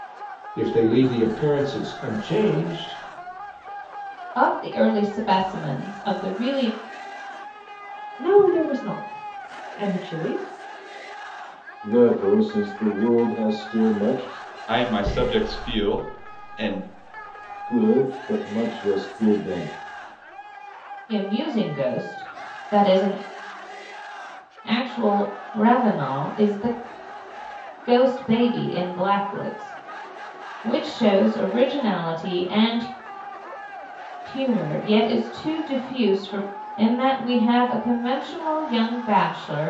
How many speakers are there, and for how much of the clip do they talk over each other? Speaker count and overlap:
5, no overlap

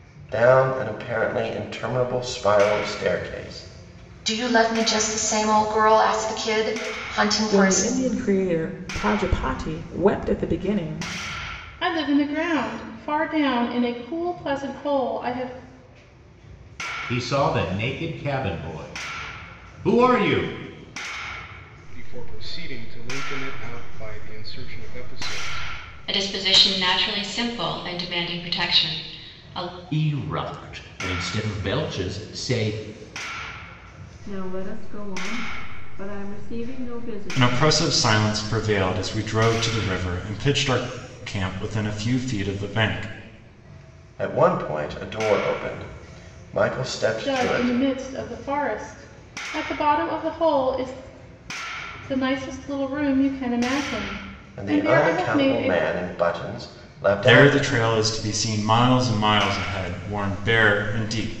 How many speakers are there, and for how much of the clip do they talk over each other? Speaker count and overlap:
10, about 6%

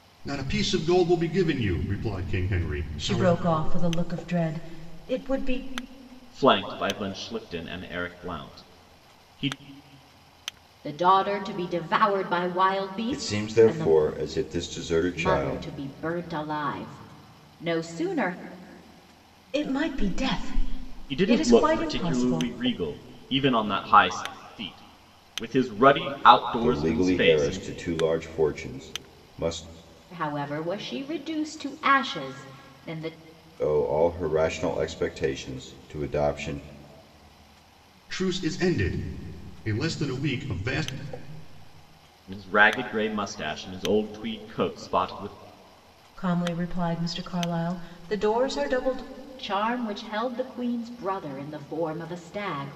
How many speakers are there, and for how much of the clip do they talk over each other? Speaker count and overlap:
5, about 8%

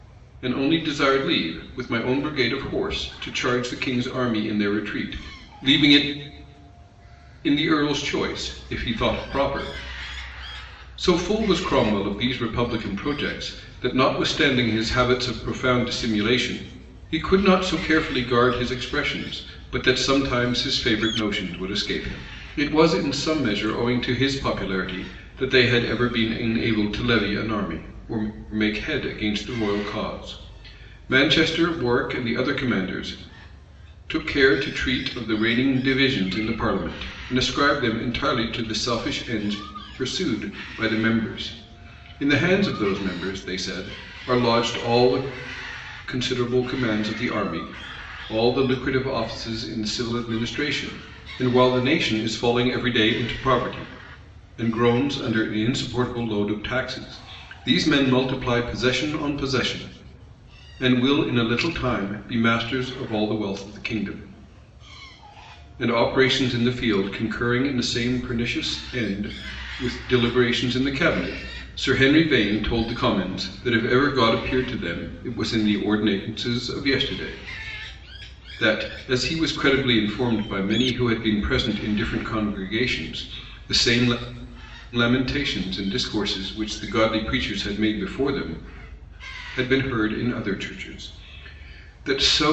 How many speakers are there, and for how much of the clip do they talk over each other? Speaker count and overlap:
1, no overlap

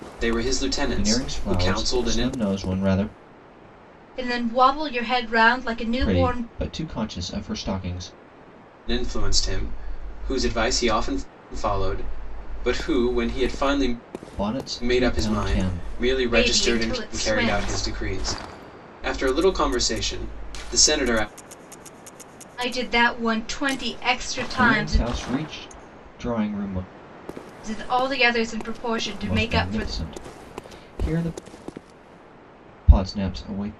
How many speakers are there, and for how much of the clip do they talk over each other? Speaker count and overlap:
3, about 17%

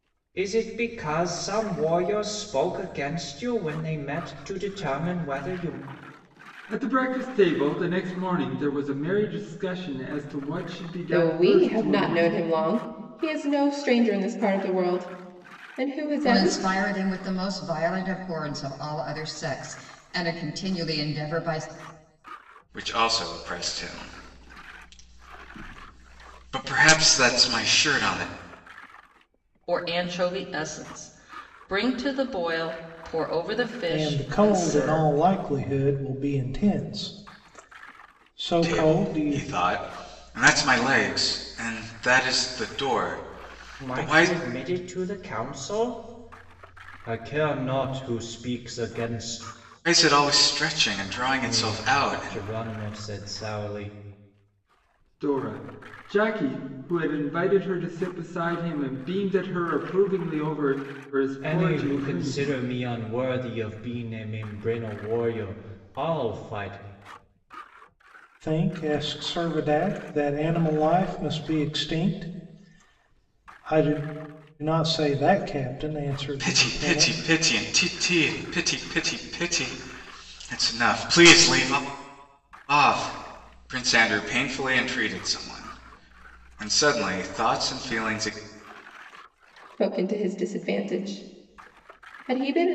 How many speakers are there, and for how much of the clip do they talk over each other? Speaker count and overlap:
7, about 8%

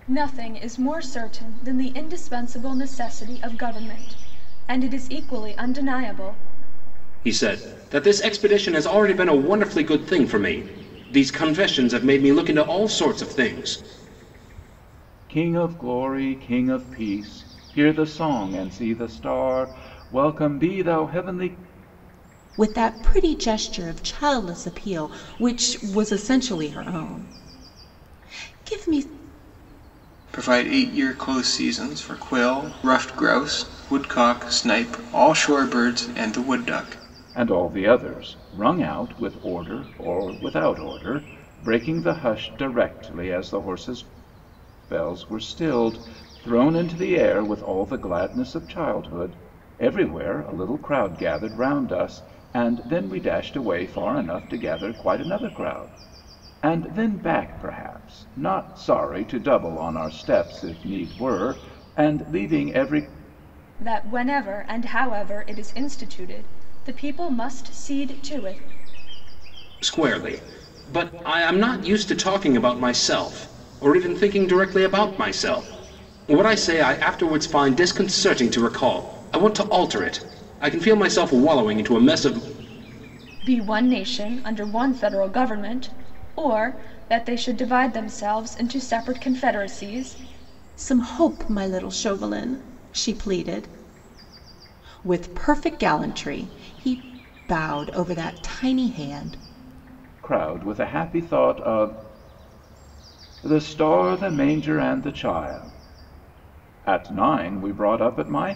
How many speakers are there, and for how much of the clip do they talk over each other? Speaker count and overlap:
5, no overlap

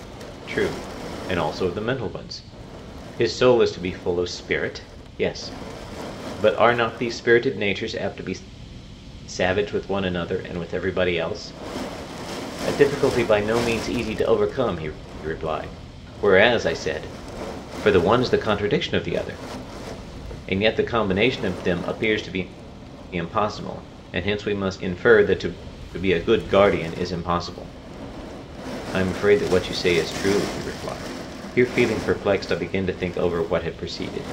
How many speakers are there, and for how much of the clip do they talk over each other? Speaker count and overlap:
1, no overlap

